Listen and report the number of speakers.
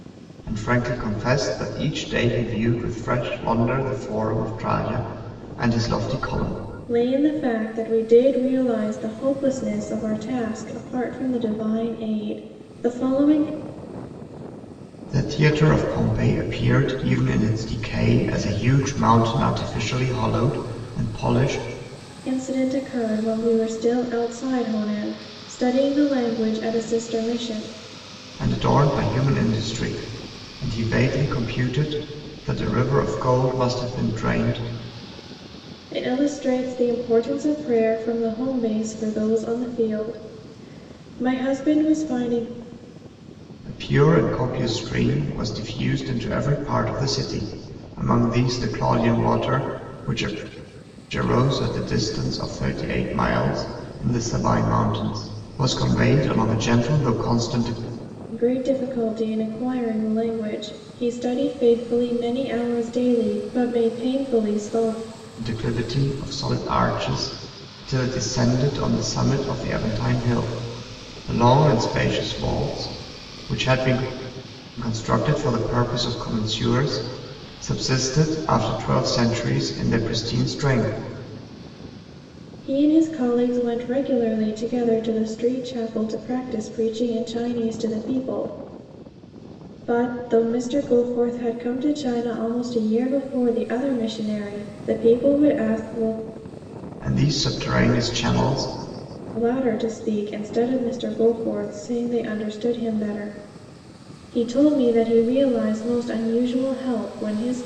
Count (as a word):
two